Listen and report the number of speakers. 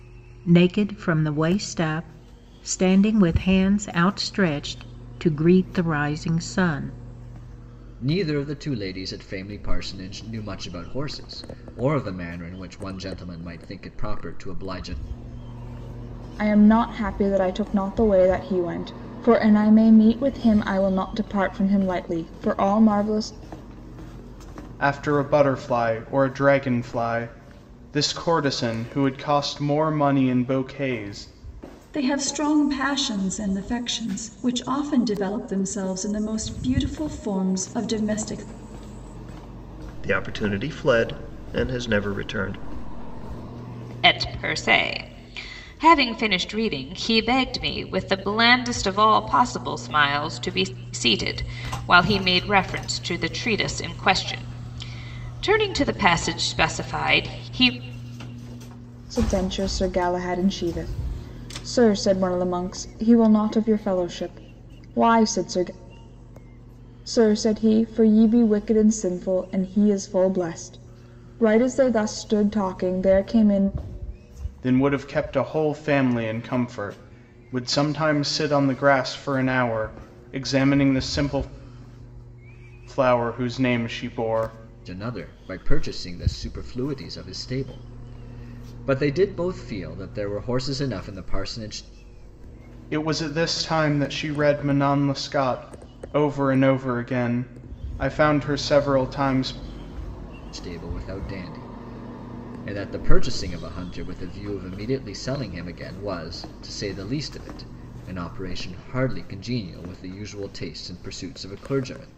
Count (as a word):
seven